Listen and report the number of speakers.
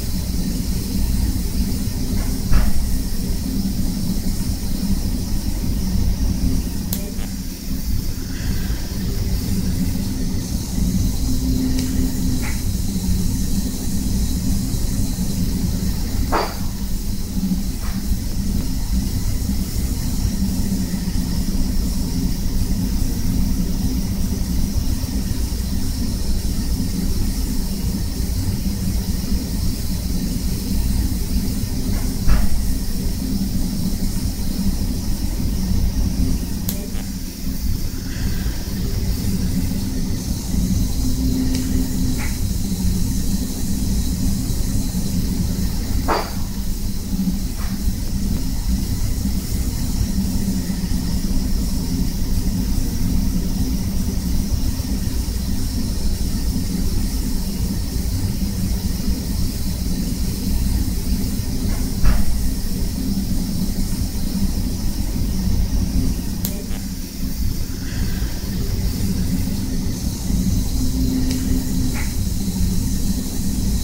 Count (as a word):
zero